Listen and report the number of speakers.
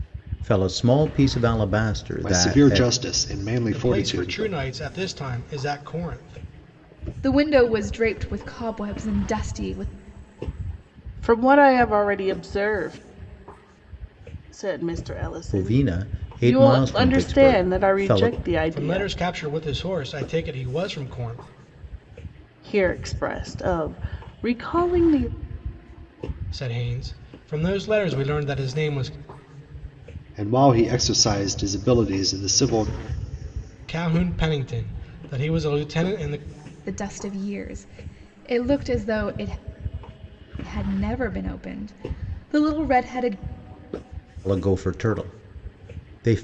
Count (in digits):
5